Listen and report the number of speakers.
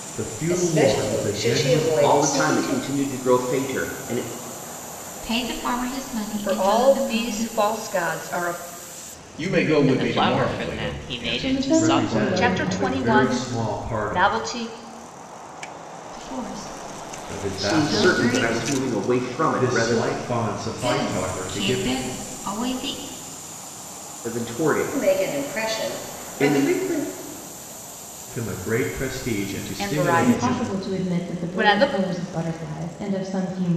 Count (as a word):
eight